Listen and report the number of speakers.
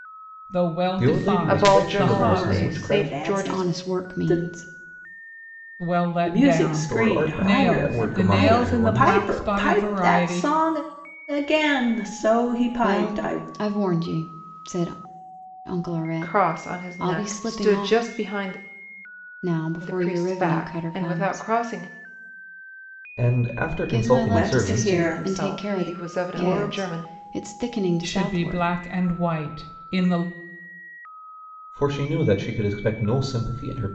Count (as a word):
five